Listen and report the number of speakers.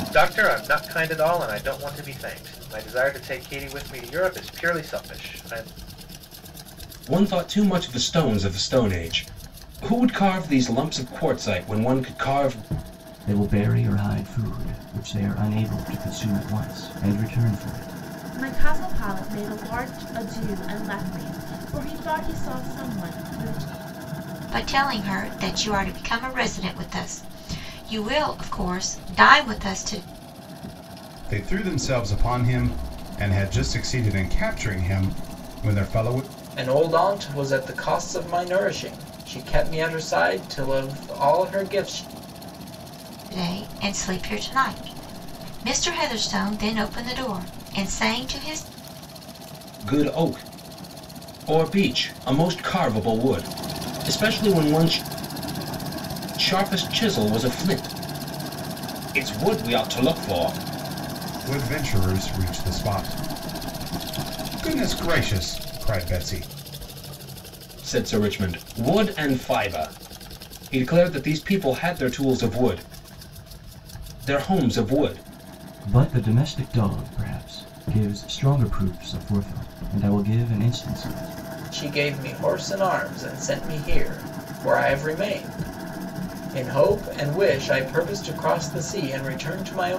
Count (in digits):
7